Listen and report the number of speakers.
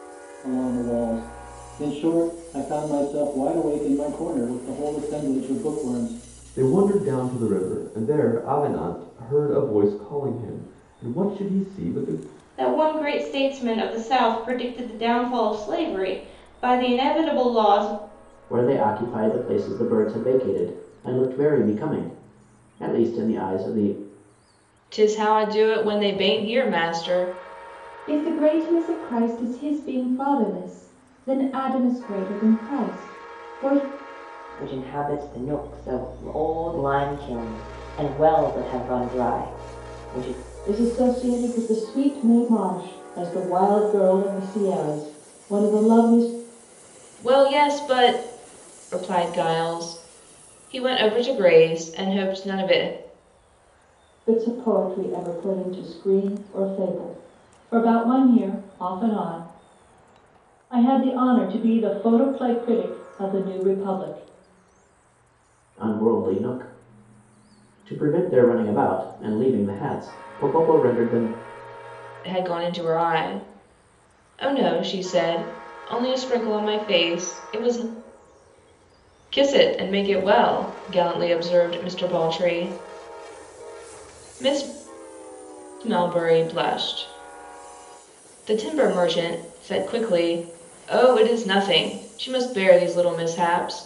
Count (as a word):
eight